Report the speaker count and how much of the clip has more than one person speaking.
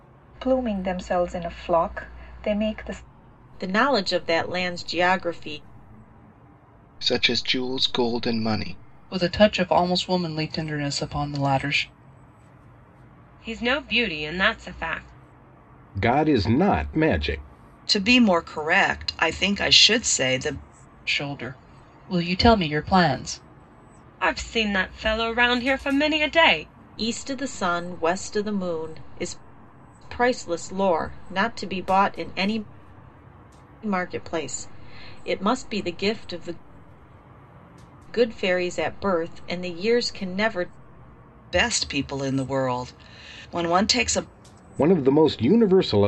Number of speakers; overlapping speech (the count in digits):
7, no overlap